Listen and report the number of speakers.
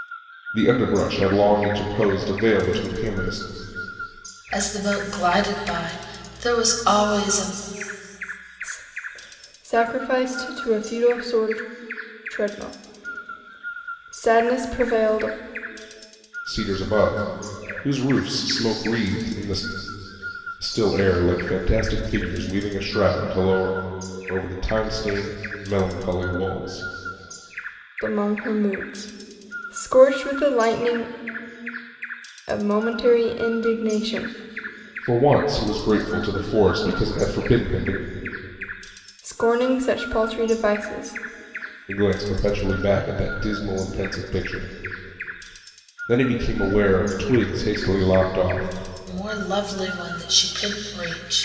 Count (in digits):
3